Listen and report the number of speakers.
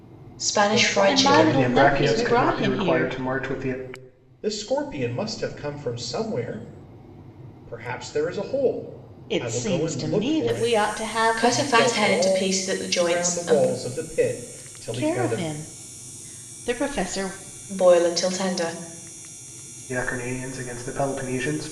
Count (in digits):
4